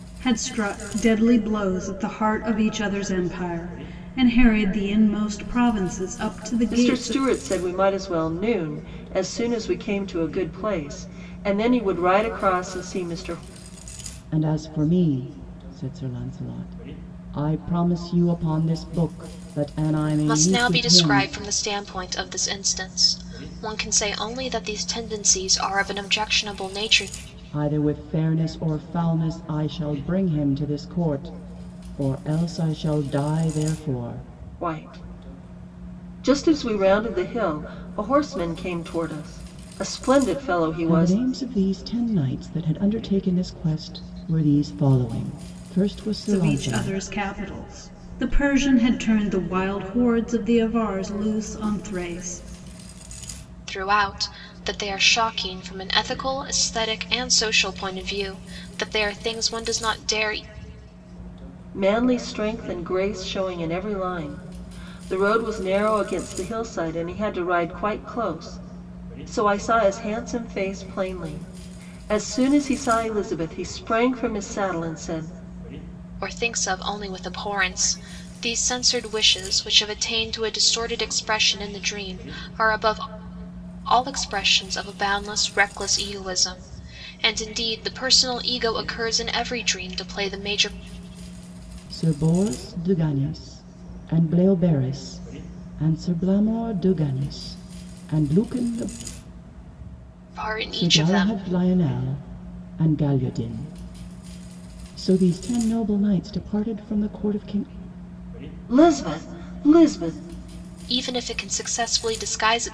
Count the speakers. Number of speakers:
four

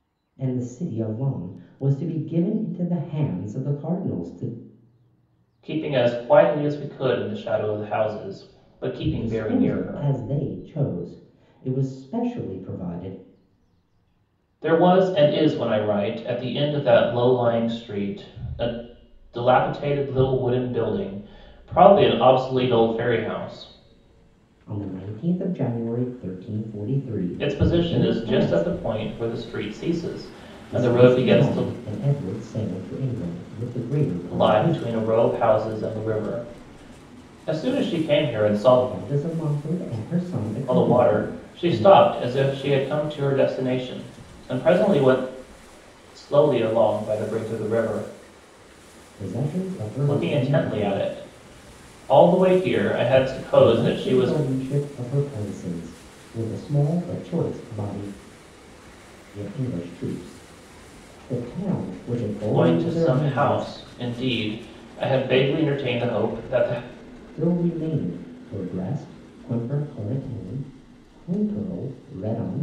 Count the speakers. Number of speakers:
two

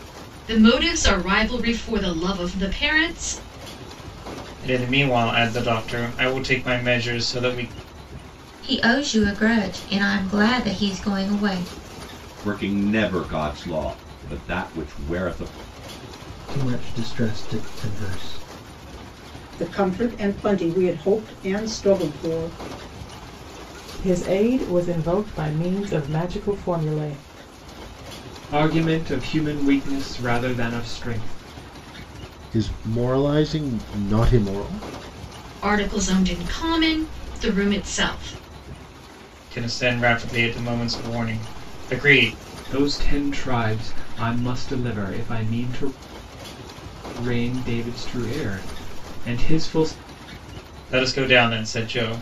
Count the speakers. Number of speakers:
nine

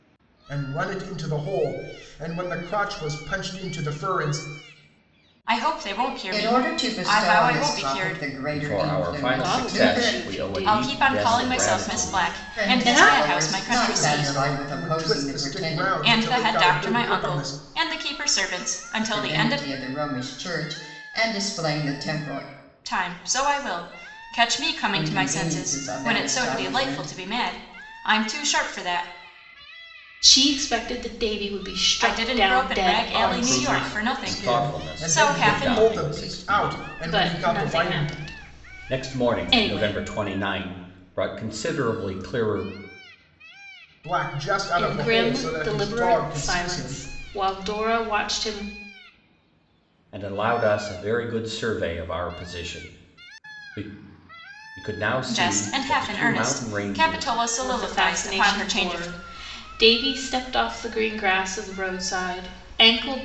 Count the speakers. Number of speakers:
five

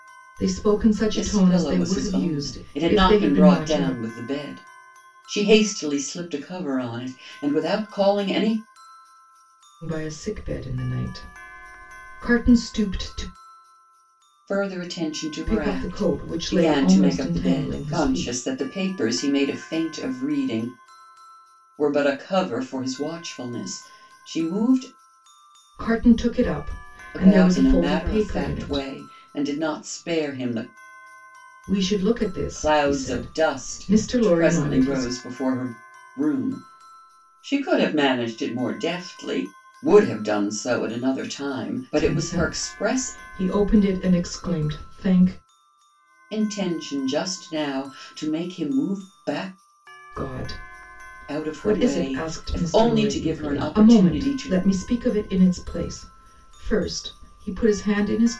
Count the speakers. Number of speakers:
two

